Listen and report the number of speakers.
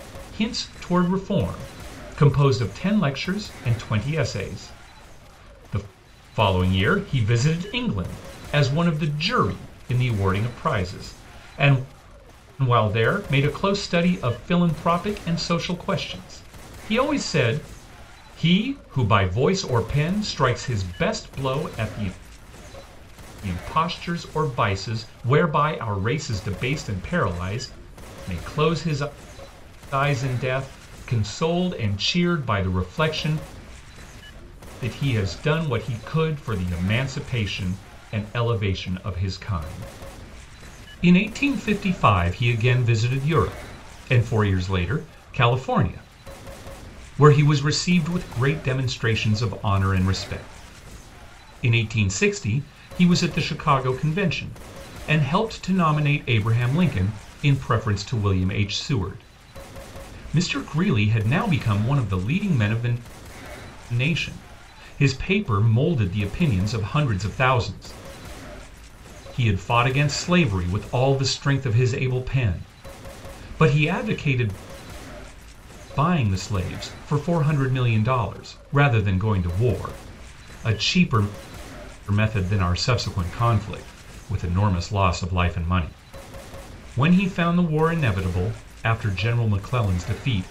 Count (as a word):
one